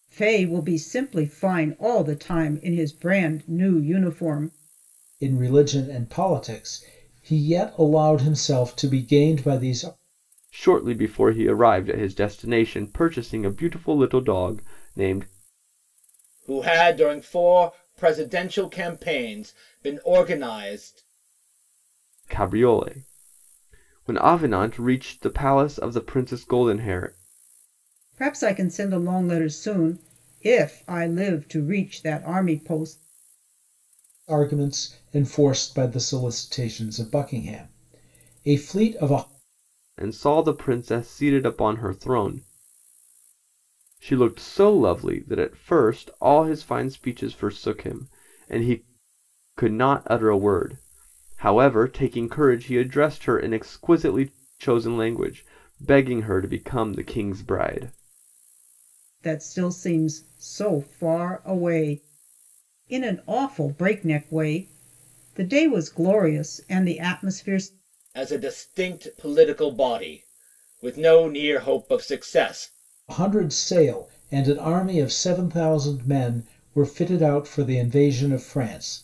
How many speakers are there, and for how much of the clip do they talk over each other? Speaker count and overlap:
4, no overlap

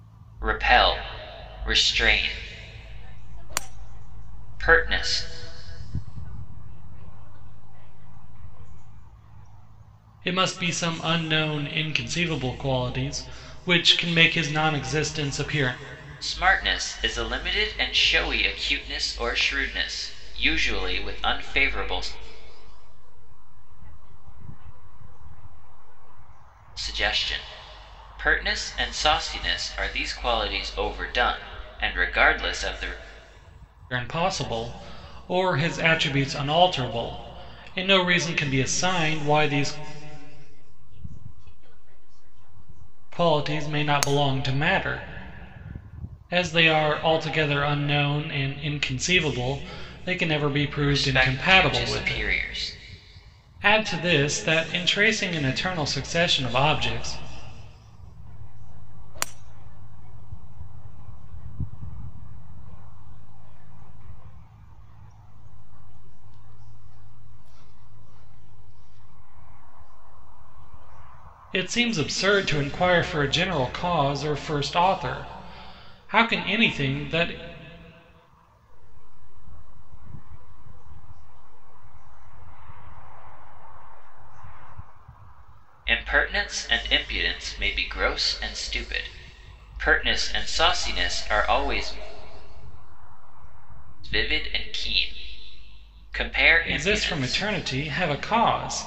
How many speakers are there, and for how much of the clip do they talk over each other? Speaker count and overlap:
3, about 15%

